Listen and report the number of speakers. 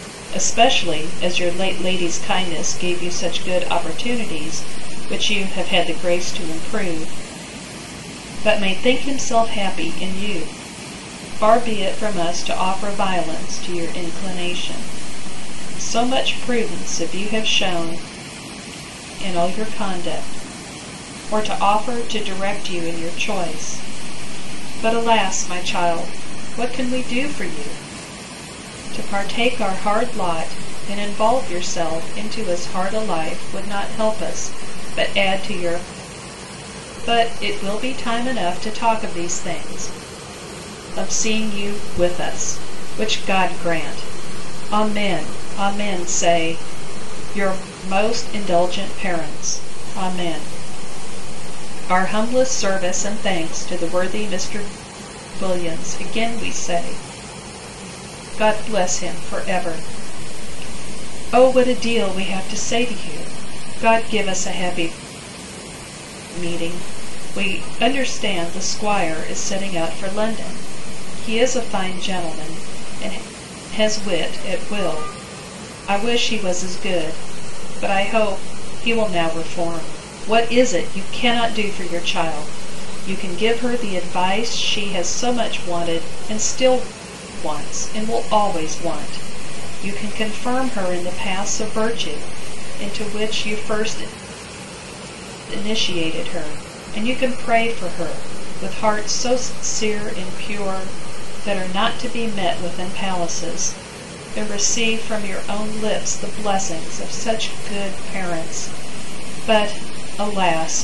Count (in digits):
1